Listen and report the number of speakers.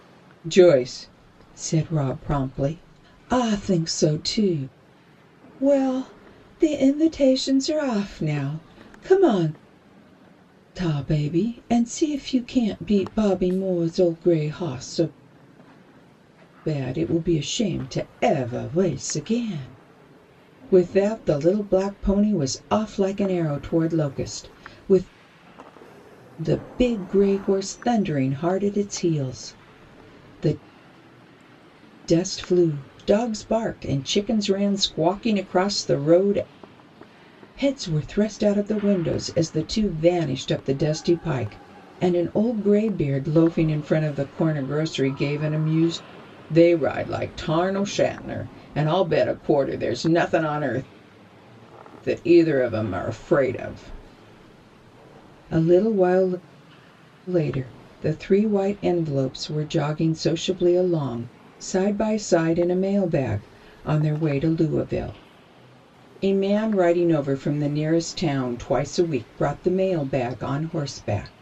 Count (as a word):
one